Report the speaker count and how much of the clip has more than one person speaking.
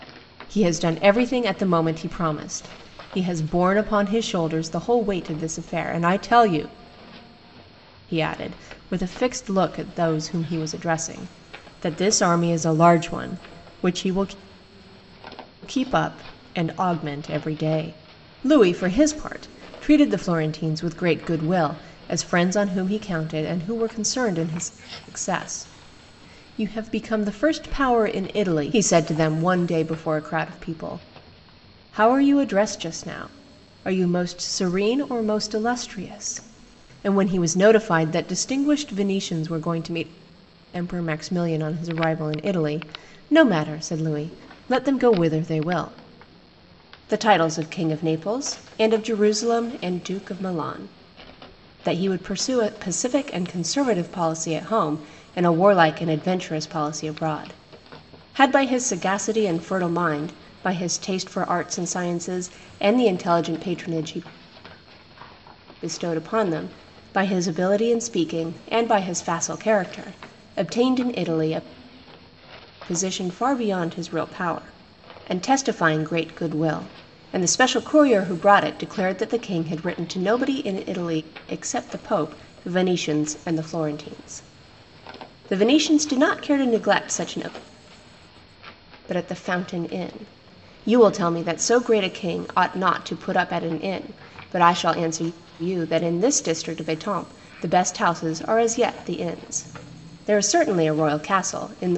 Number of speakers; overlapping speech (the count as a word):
one, no overlap